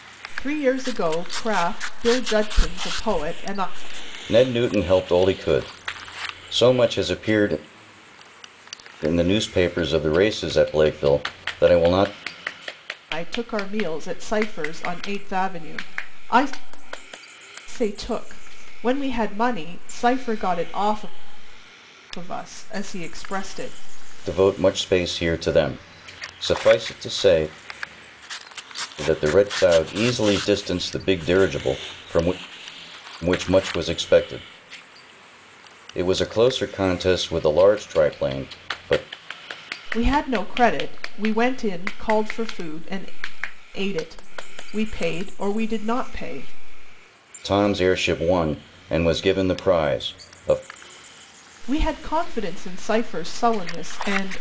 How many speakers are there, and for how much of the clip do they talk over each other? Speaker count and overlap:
two, no overlap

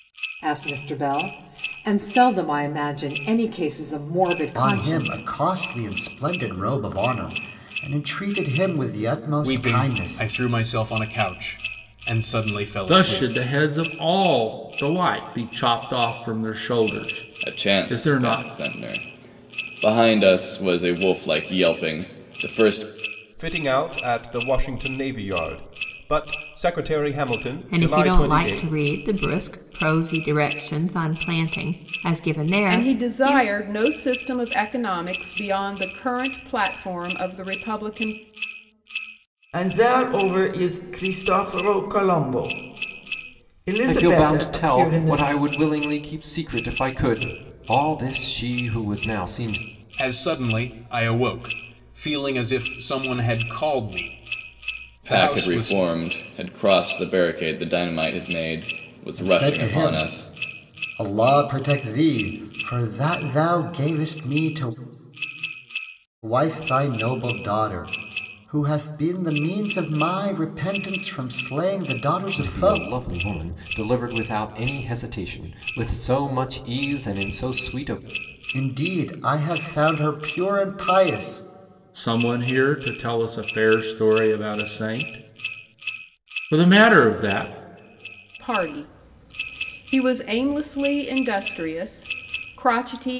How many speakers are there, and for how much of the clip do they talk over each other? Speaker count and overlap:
ten, about 10%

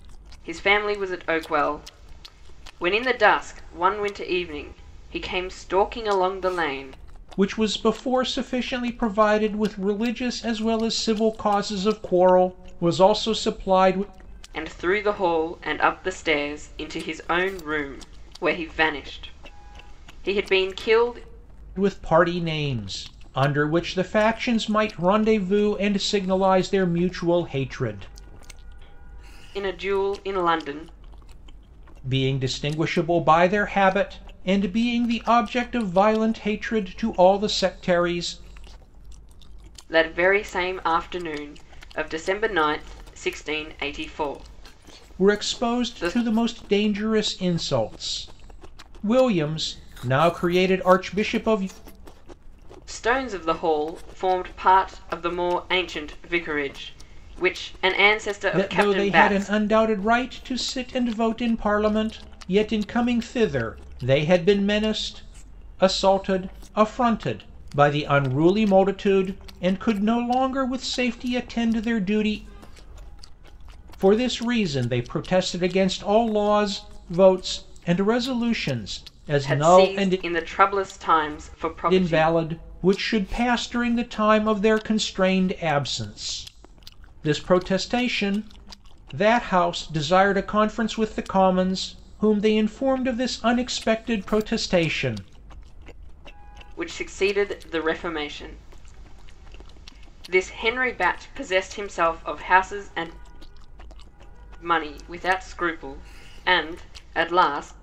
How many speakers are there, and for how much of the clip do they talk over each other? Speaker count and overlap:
two, about 3%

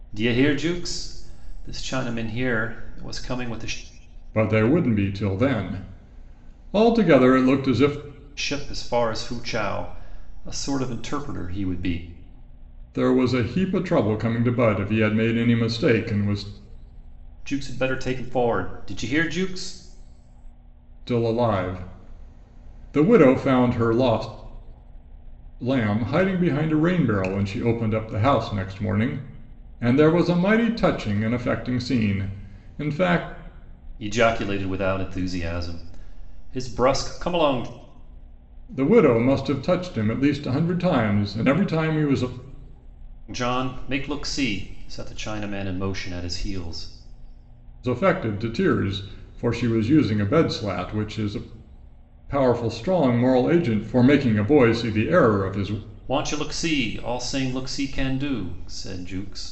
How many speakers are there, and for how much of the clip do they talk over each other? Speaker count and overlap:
two, no overlap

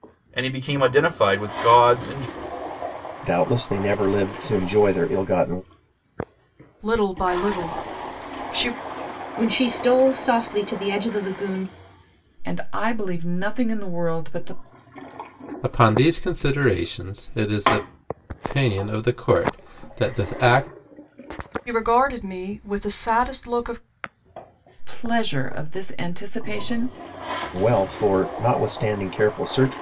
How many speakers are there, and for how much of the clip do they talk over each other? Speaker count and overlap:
six, no overlap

